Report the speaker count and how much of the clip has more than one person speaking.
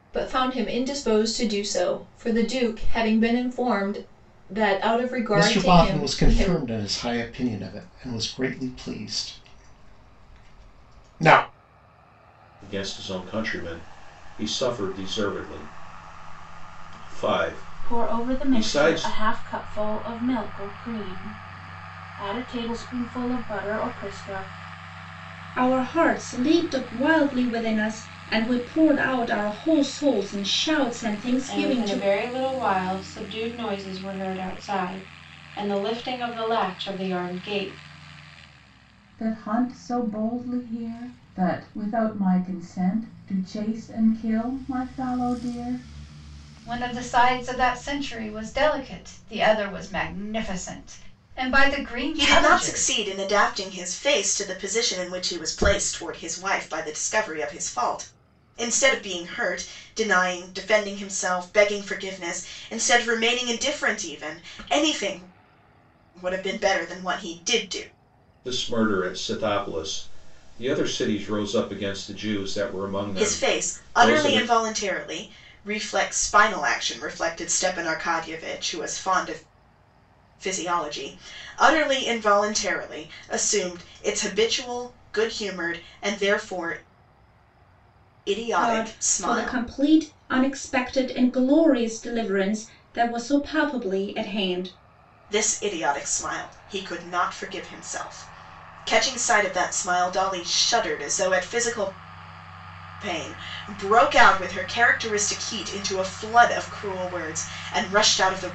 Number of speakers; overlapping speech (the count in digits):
9, about 6%